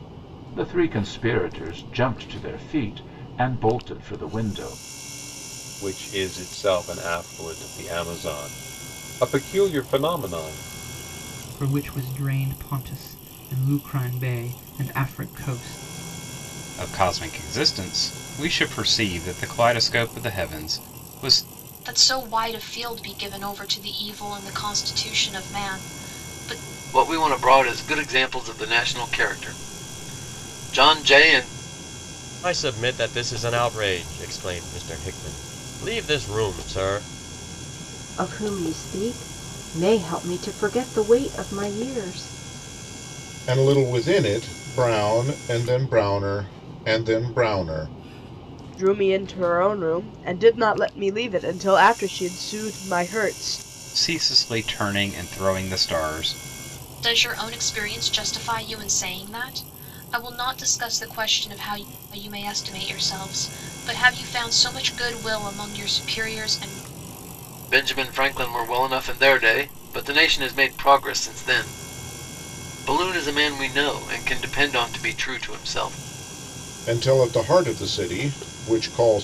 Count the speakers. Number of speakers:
ten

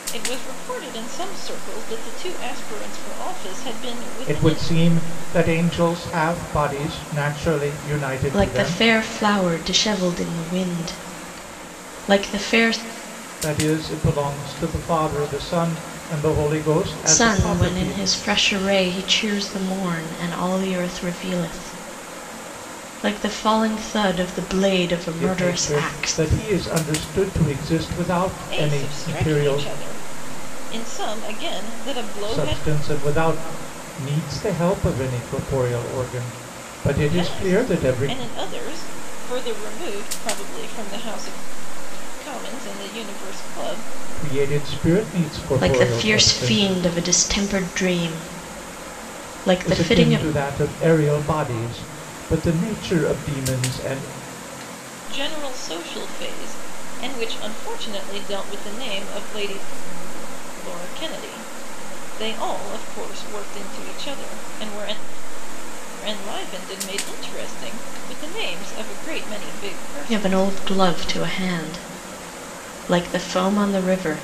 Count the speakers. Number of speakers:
three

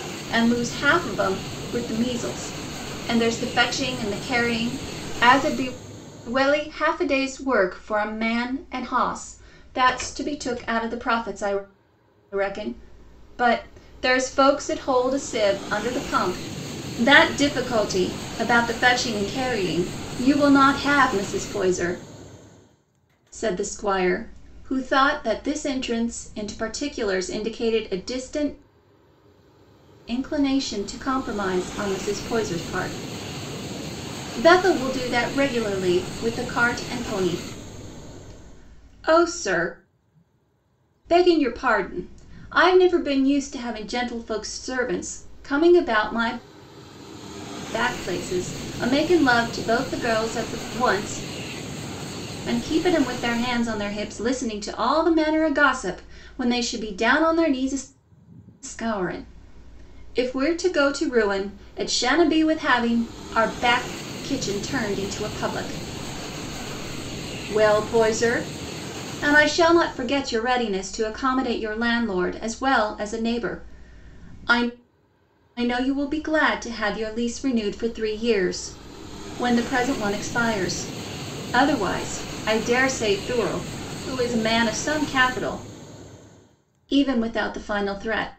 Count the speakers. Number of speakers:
one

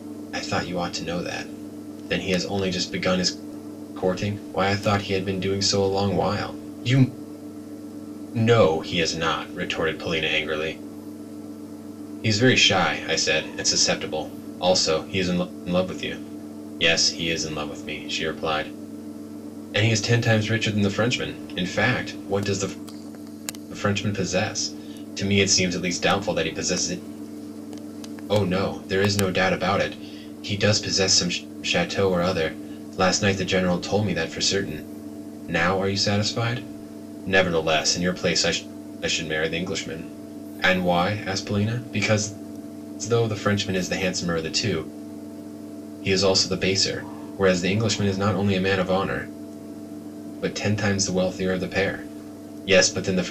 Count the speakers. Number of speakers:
one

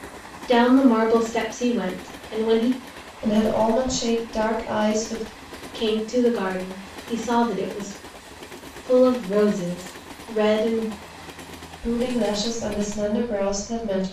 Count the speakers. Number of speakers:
two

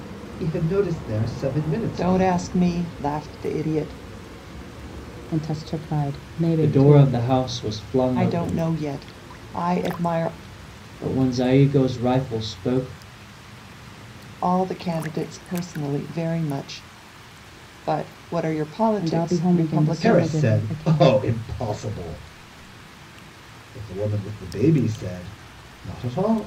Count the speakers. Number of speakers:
four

